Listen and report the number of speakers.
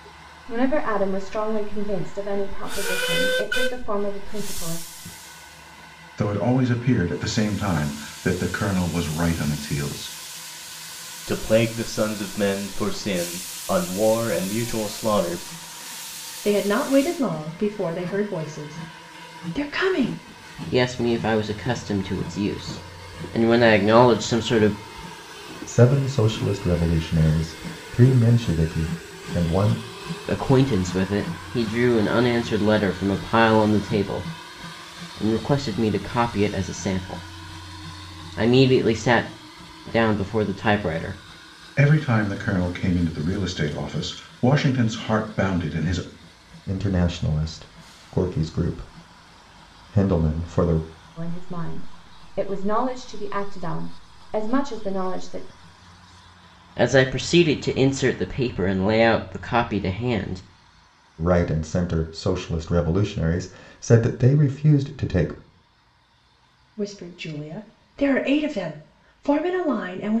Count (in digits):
6